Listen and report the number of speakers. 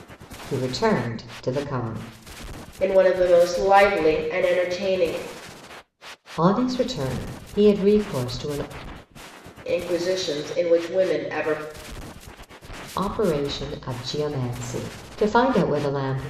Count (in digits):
2